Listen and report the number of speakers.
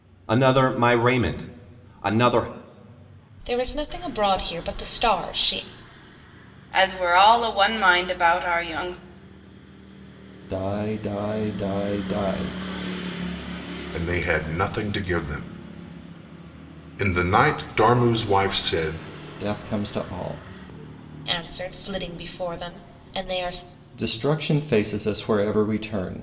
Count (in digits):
5